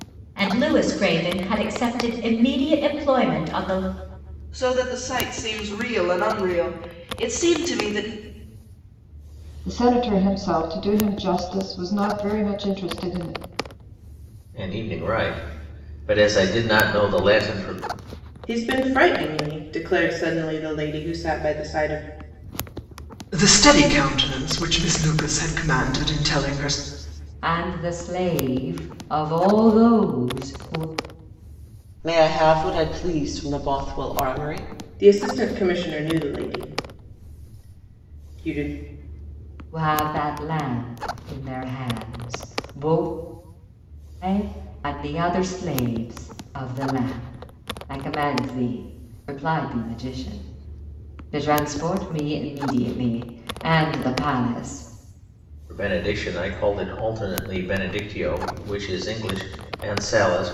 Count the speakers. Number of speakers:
eight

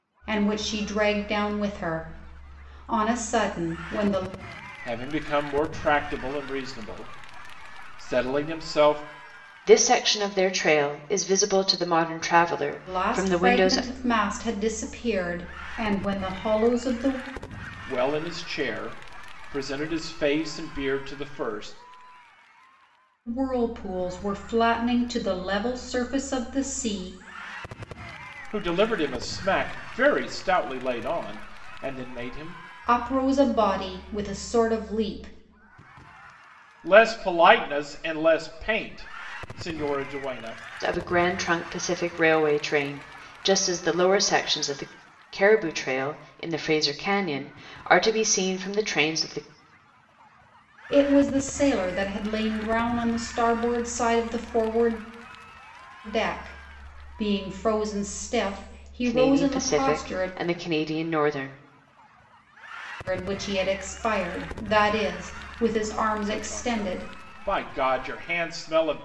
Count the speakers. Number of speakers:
three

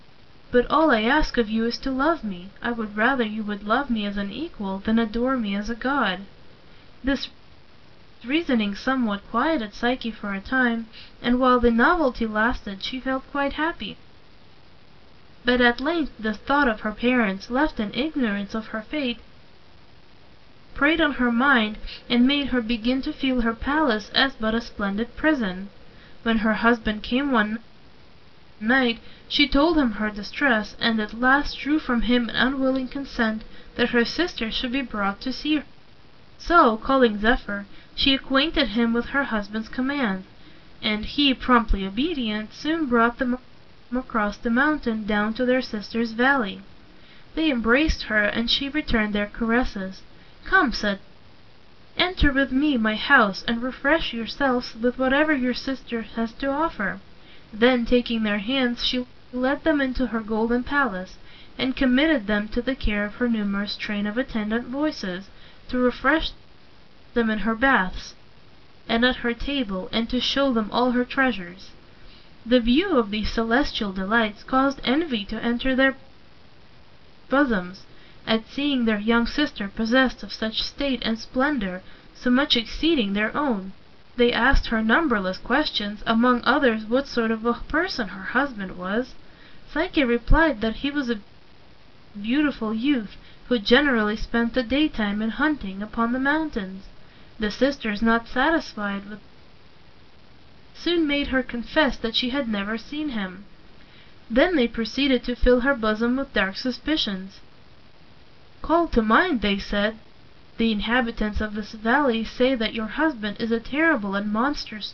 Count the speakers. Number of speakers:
one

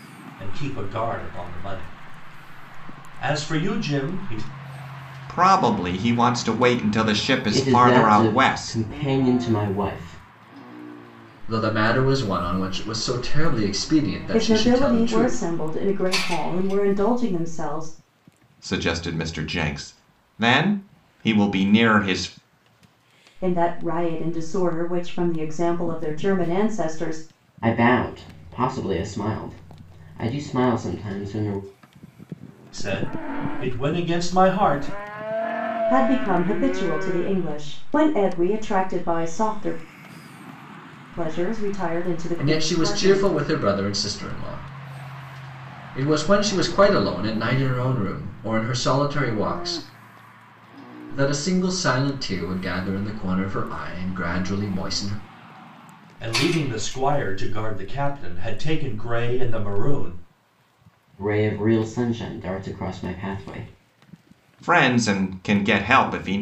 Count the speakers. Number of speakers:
five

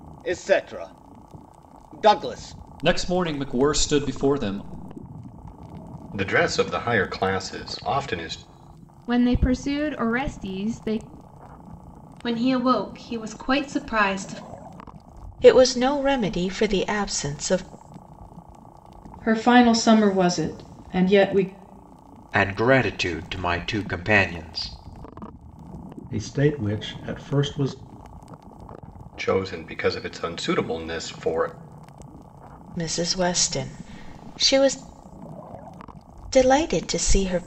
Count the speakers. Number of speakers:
nine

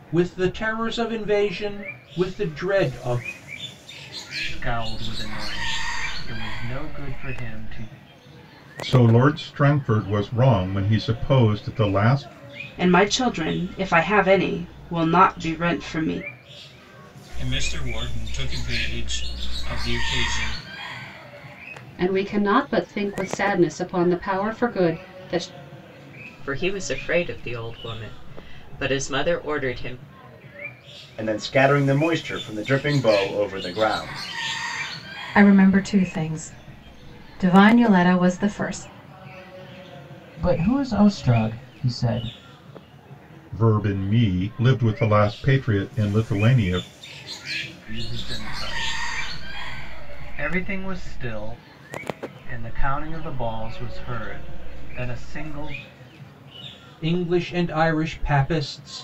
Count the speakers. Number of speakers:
ten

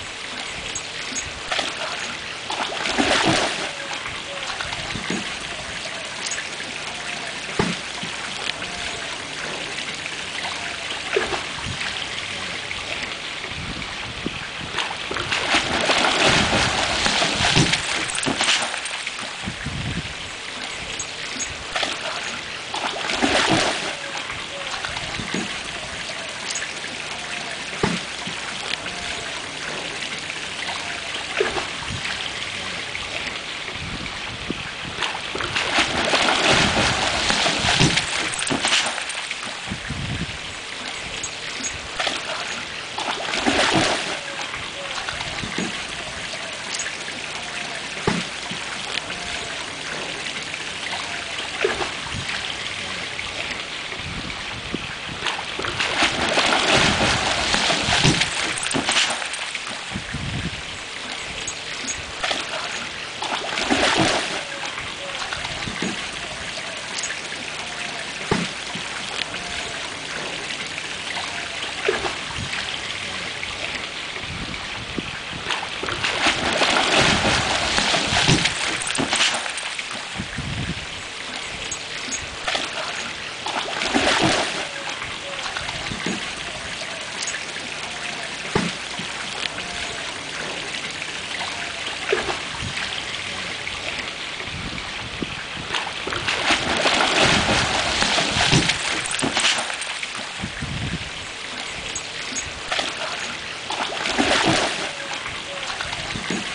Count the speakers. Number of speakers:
zero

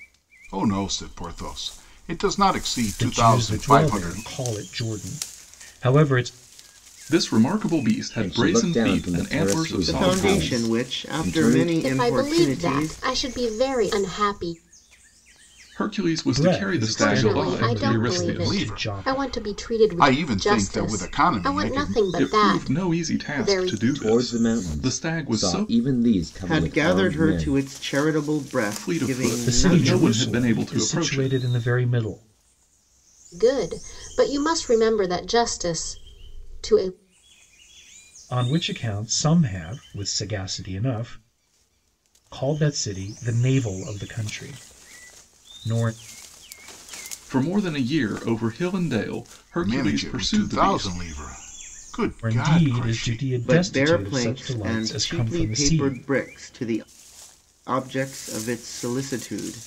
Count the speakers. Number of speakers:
six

